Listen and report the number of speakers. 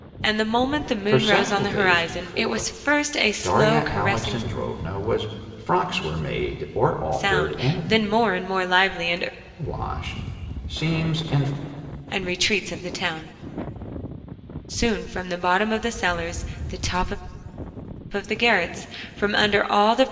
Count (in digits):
2